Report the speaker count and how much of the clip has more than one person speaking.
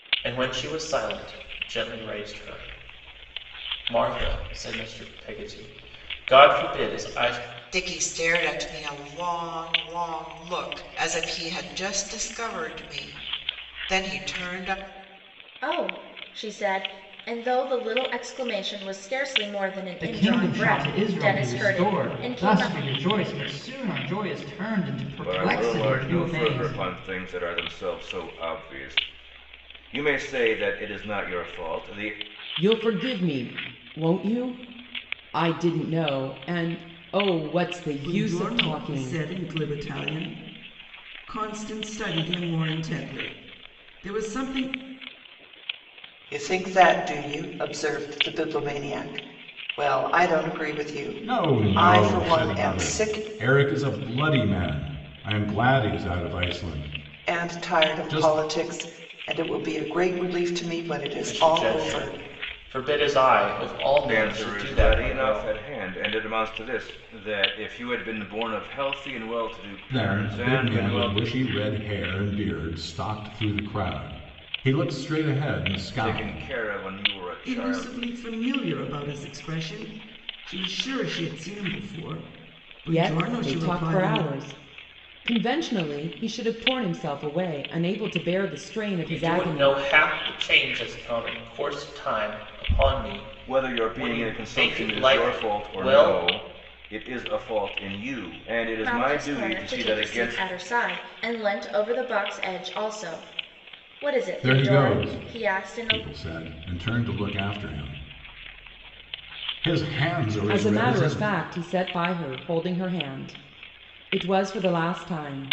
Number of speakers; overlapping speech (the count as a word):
nine, about 20%